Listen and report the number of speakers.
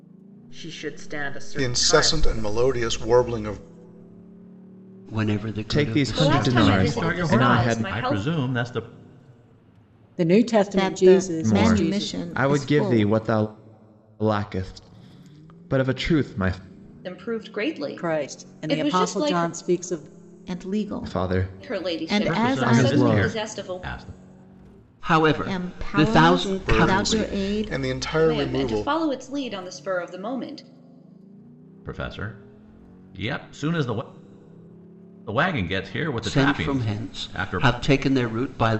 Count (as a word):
eight